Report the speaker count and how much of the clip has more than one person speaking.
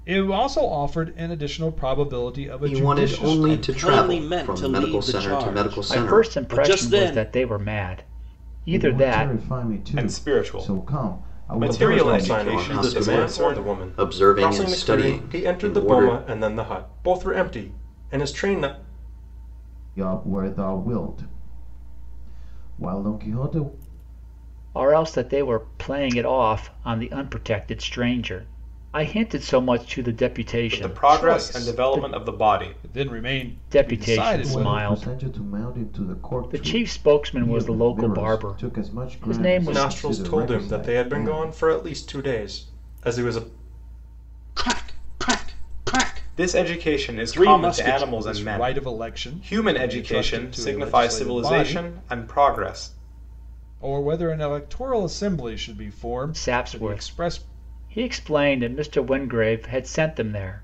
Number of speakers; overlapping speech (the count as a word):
seven, about 43%